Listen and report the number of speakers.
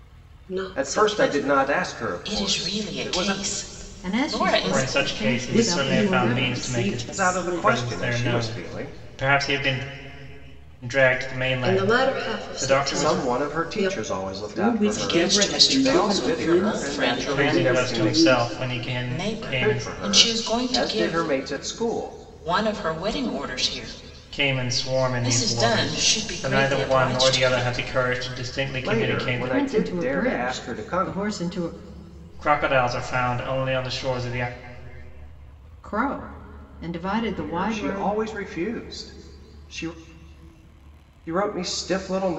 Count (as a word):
six